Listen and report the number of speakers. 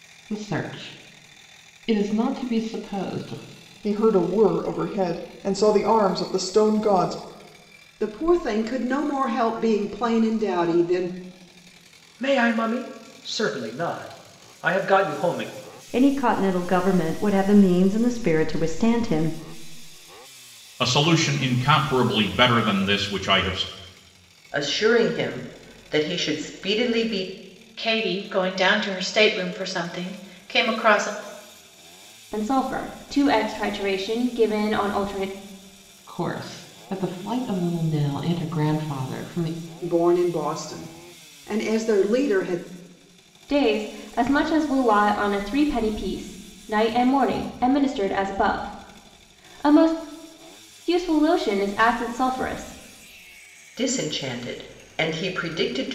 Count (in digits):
9